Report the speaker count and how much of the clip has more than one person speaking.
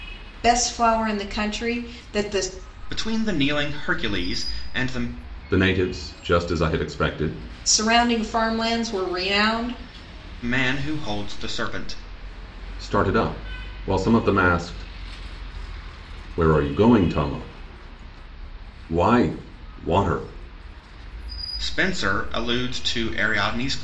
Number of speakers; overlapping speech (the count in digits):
3, no overlap